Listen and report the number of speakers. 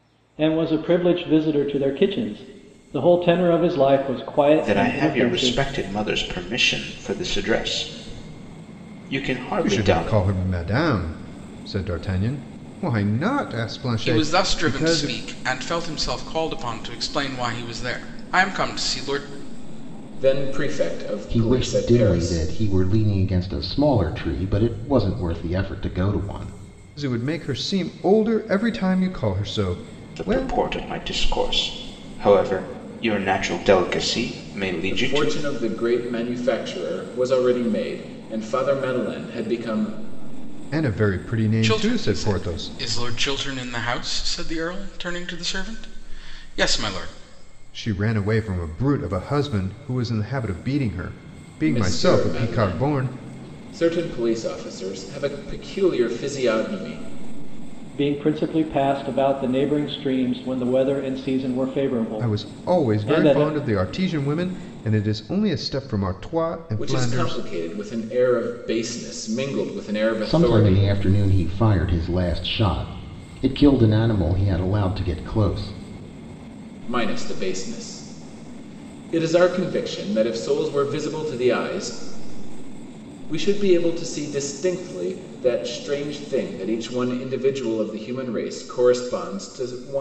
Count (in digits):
6